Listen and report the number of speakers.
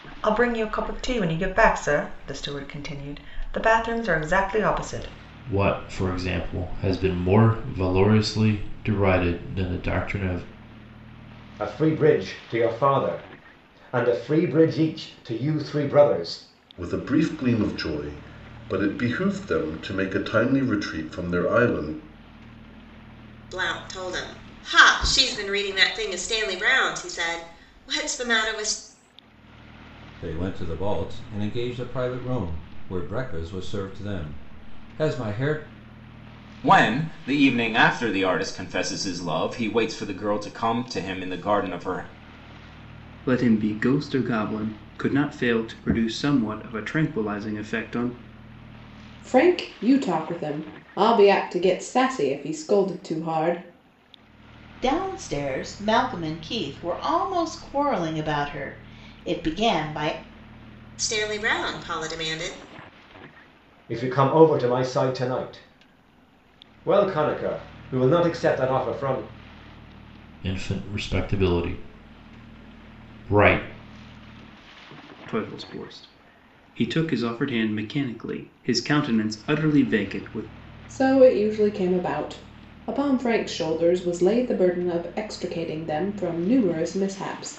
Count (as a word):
ten